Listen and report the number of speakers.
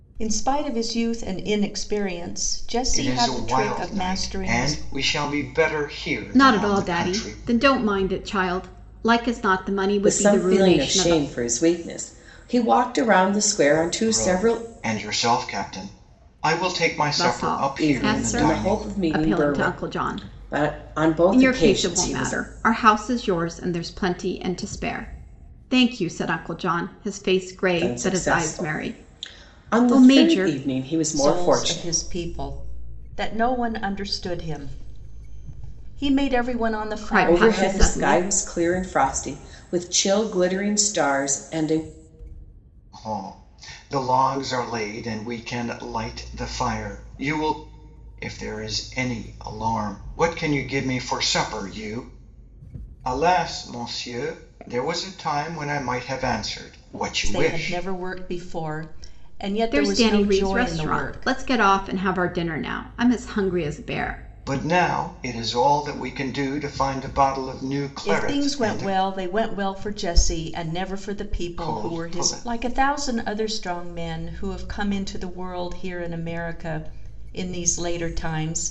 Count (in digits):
4